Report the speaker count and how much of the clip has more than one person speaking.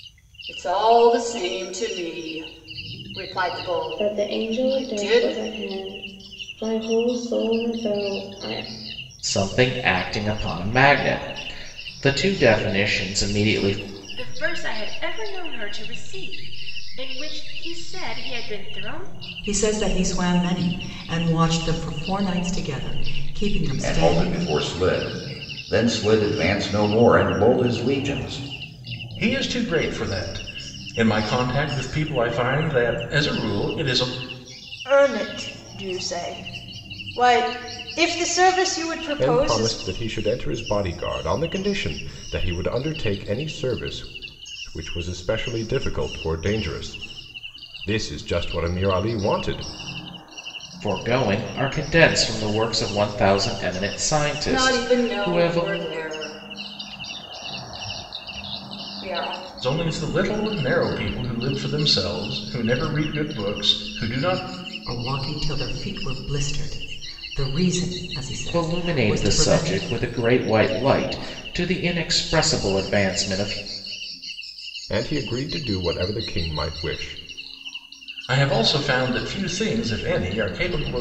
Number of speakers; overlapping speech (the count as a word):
nine, about 6%